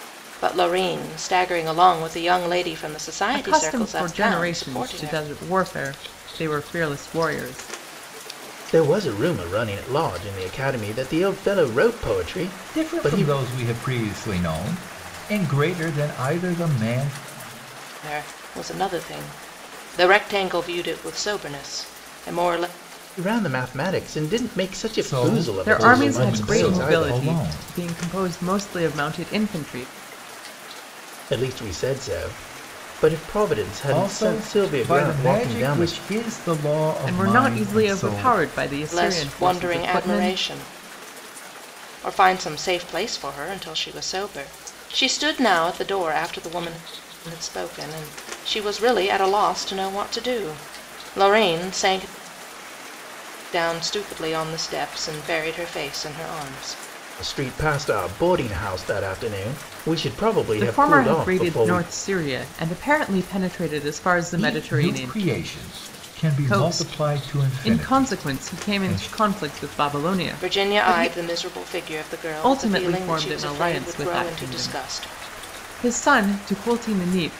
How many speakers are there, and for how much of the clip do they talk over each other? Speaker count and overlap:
4, about 24%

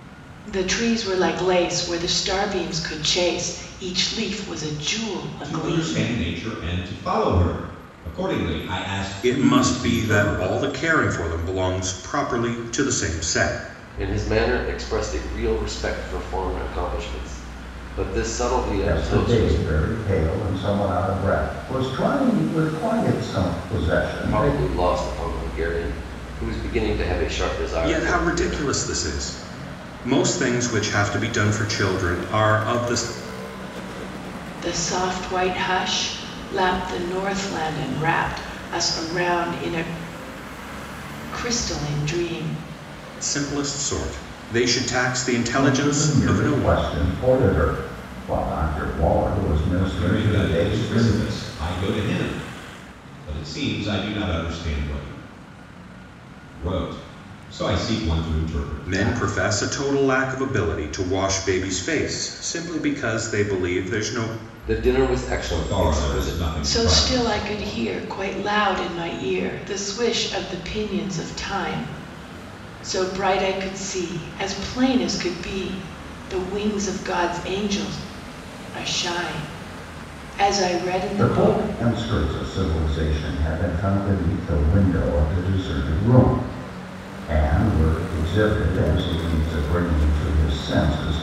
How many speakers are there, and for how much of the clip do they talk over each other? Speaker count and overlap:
5, about 11%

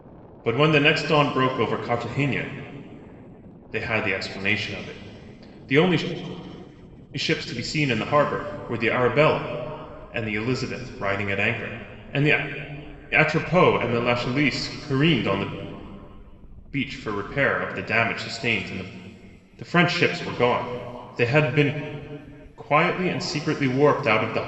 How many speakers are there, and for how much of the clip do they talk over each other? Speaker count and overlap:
1, no overlap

